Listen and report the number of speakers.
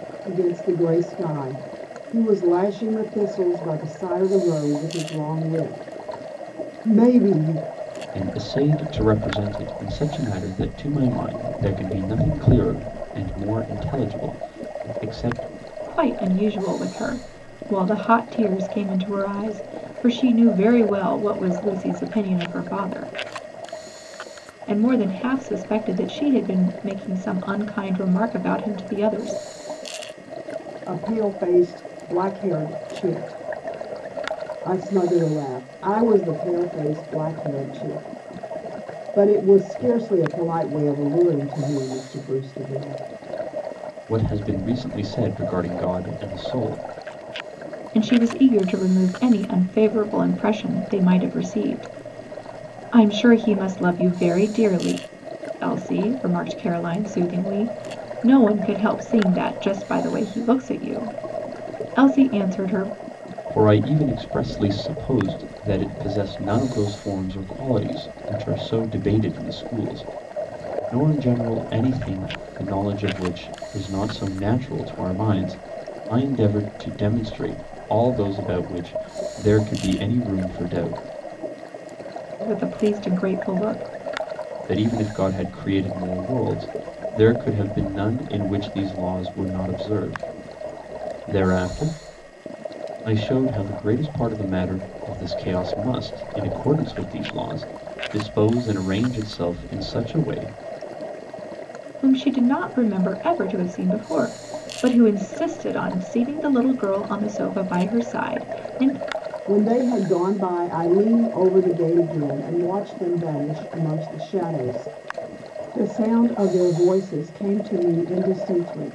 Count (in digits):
3